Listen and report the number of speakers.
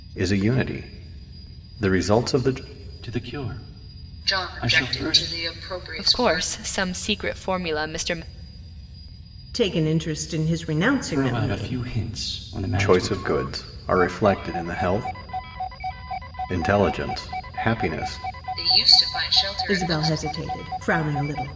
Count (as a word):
five